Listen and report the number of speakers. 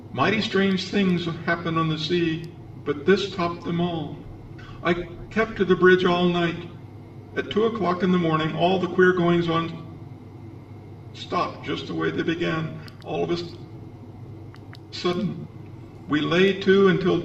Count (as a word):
one